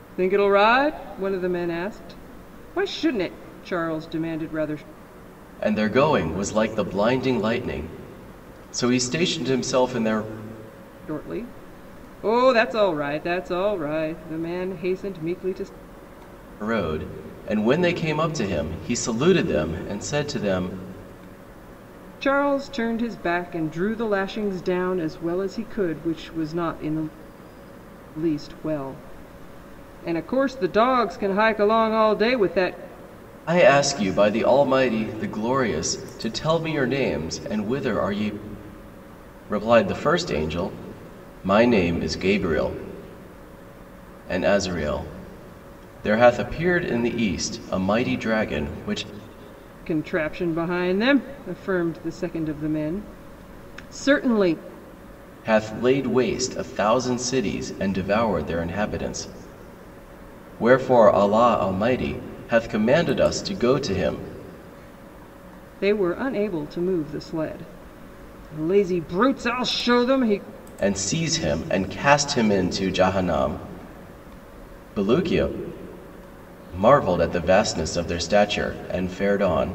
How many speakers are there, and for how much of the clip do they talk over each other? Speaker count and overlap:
2, no overlap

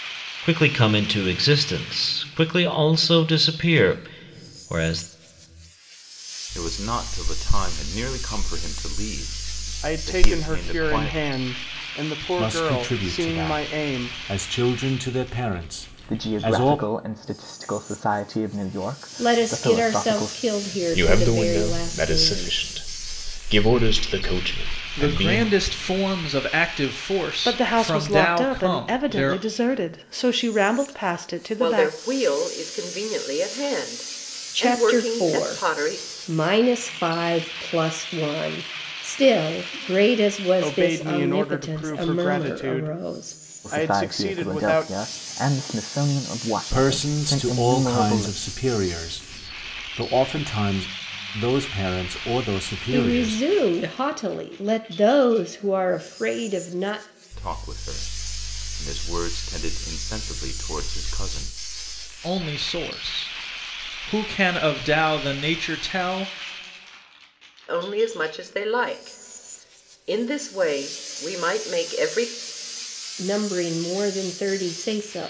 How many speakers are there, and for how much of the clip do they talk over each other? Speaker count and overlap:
10, about 24%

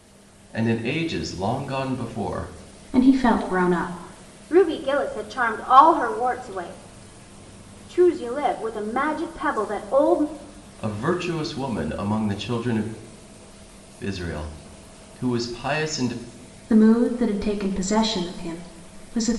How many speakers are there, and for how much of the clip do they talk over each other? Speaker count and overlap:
3, no overlap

